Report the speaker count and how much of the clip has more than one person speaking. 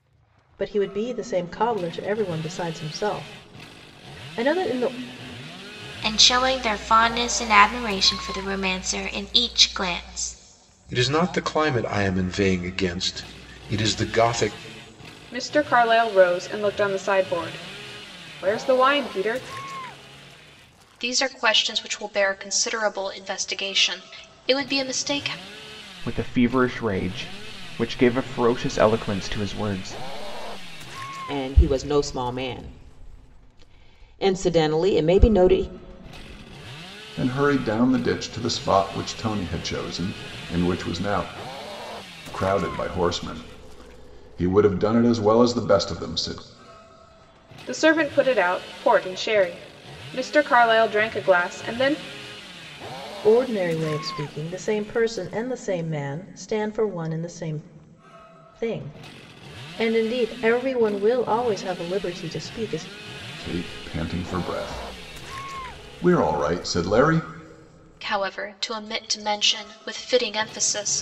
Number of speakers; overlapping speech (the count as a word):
eight, no overlap